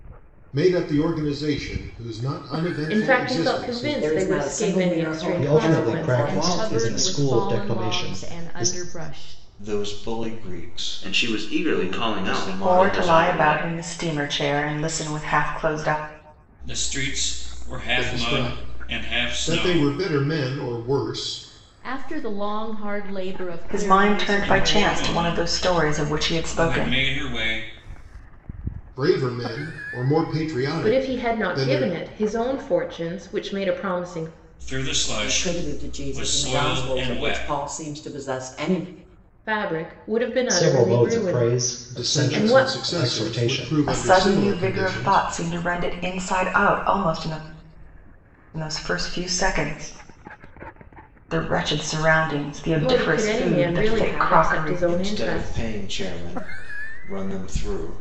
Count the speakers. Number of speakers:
9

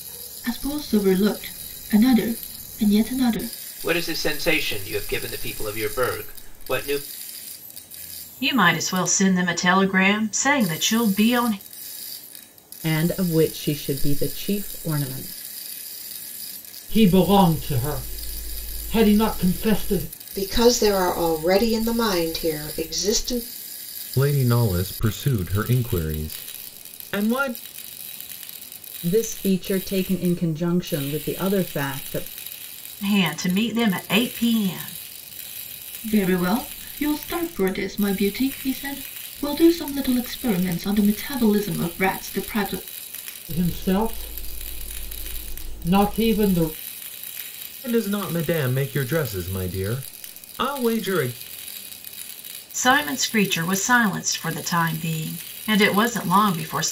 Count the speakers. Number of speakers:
7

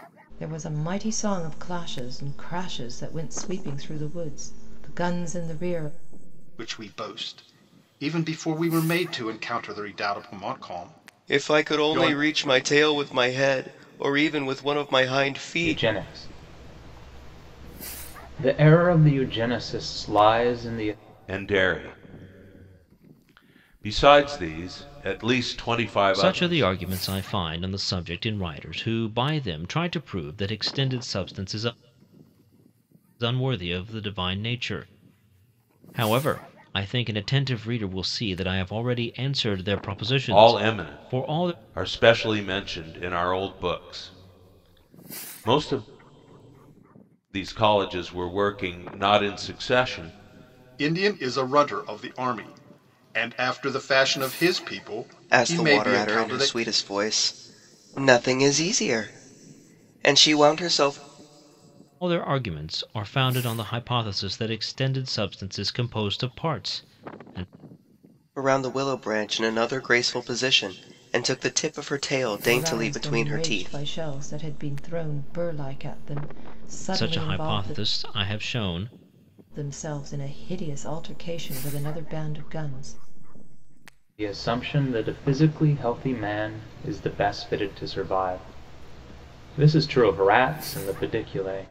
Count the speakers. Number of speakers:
6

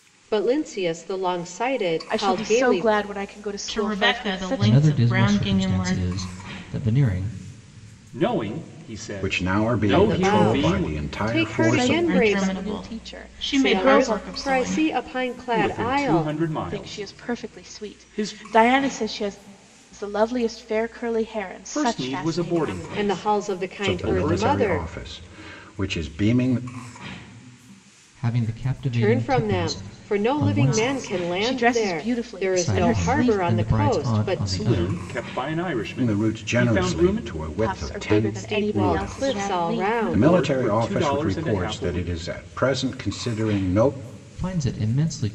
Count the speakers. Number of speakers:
6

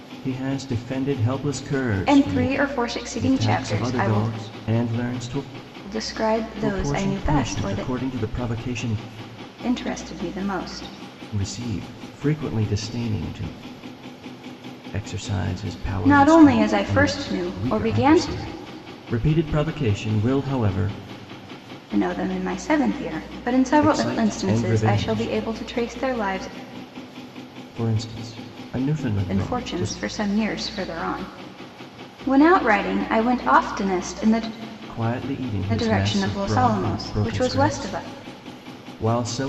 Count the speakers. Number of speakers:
2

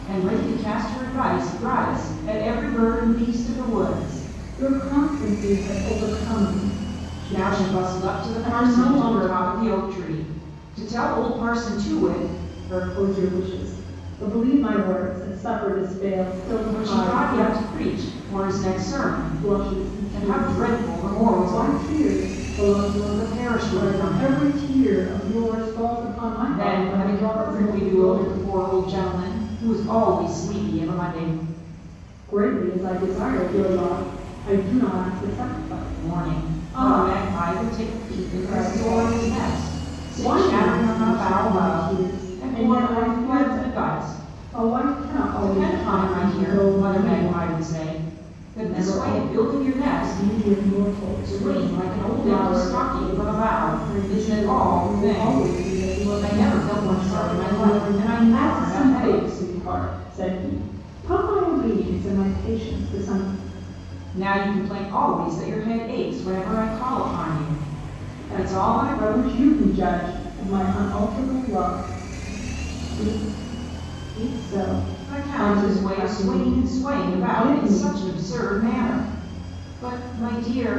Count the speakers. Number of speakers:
2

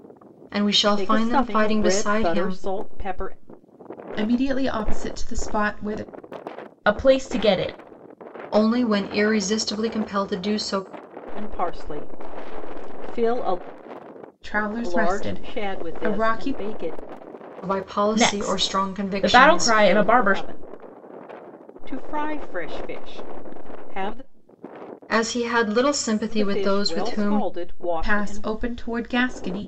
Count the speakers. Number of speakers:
4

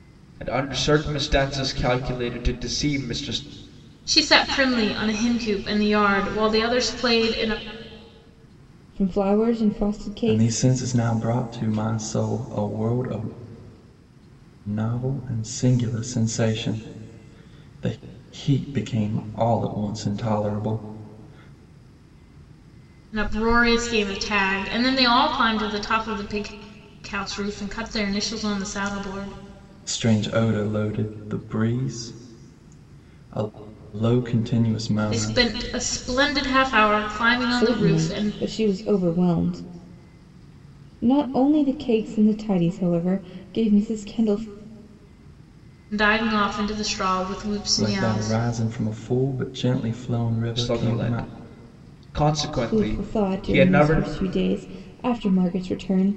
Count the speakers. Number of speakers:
4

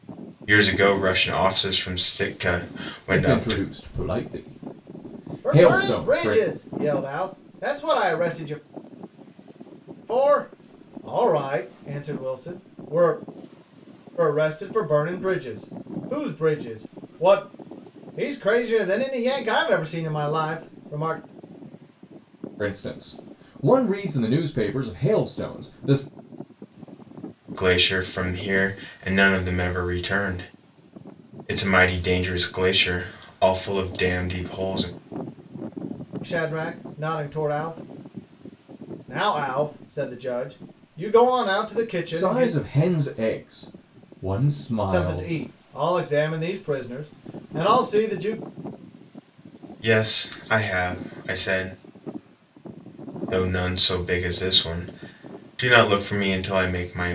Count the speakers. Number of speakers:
3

